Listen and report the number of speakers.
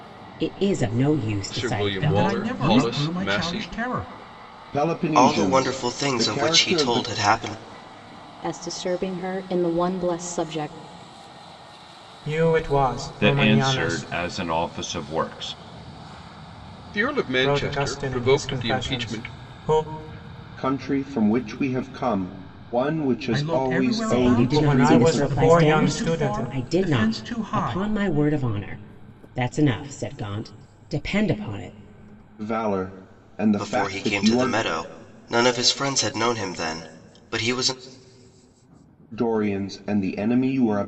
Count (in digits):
8